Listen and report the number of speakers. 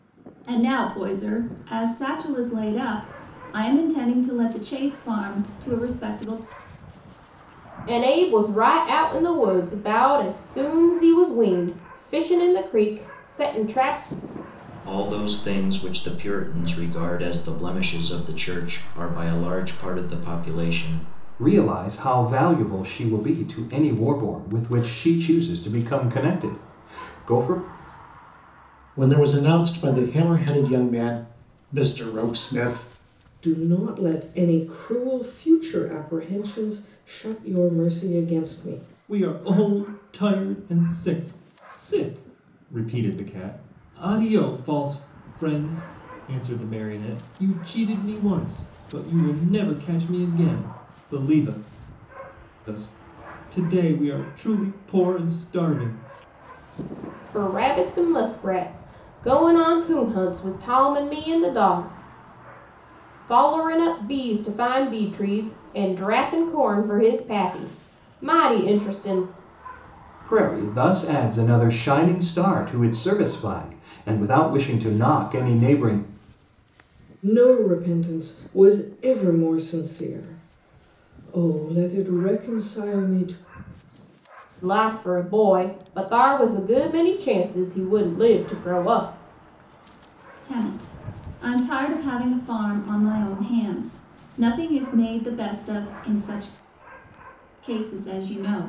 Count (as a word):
seven